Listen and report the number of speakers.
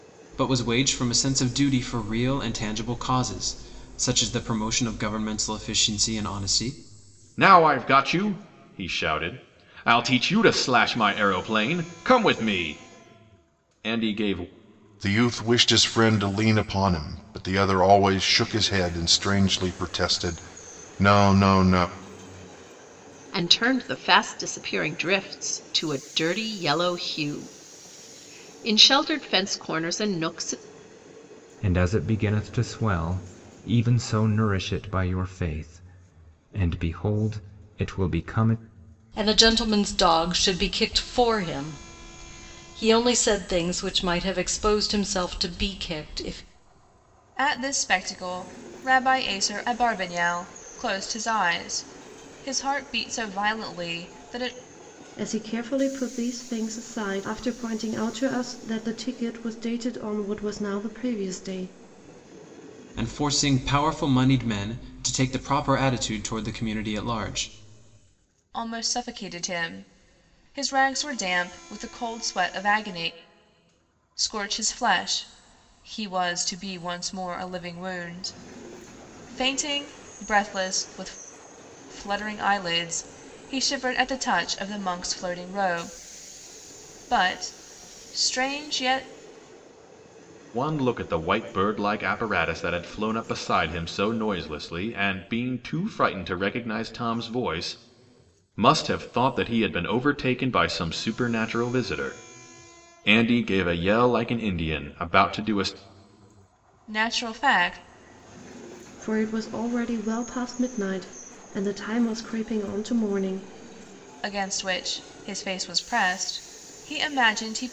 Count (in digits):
8